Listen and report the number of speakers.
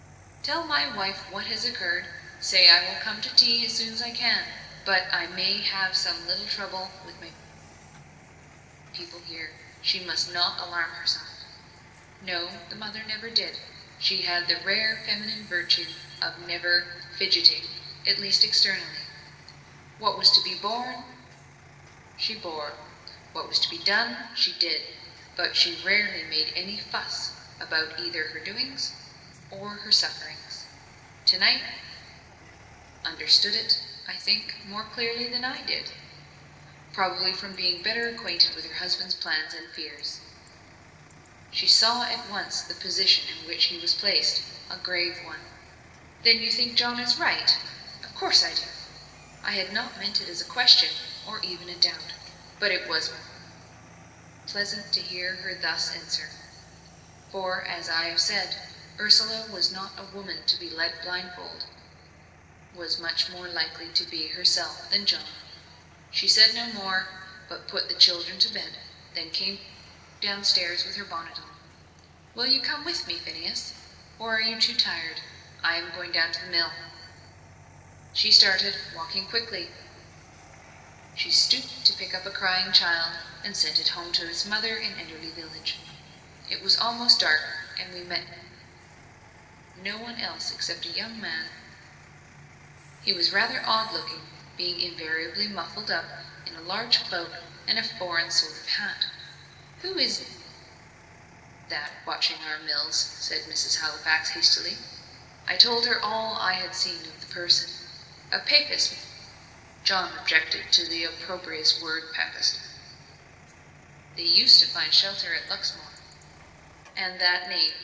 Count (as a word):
one